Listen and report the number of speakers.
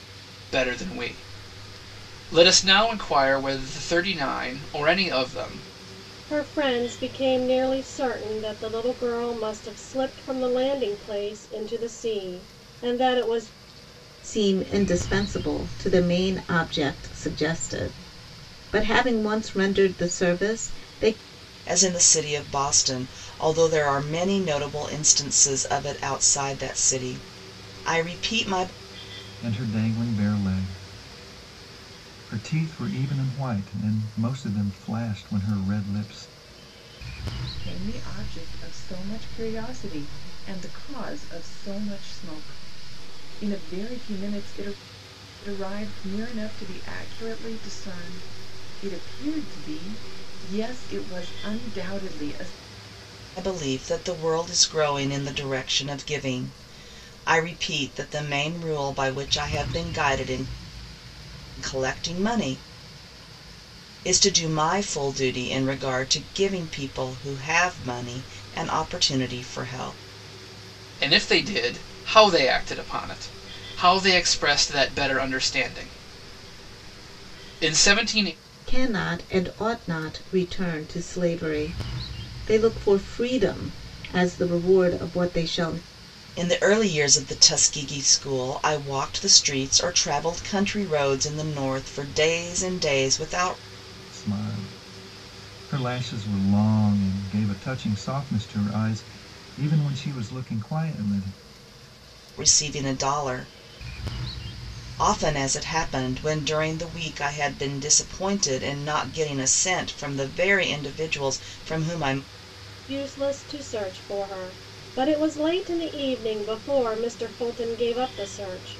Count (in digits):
6